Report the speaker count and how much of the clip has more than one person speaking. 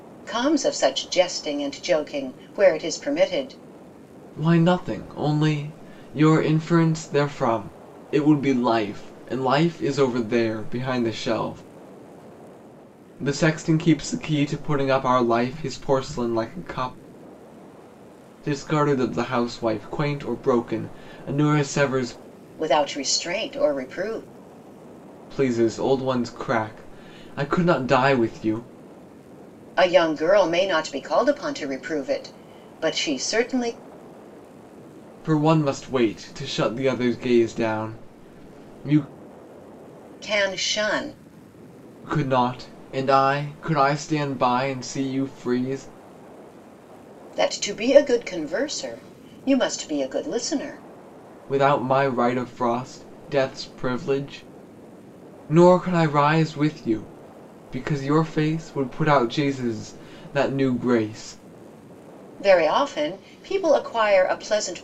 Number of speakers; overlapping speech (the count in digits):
2, no overlap